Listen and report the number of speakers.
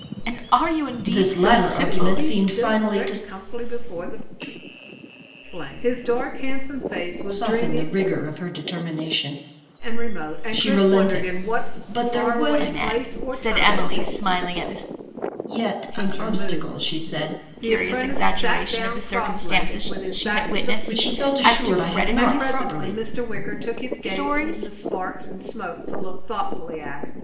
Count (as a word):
three